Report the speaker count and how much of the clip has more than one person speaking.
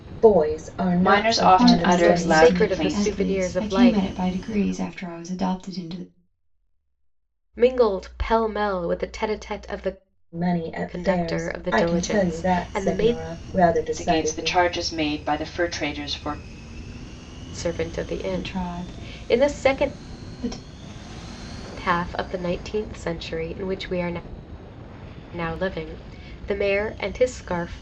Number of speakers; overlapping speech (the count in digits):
4, about 29%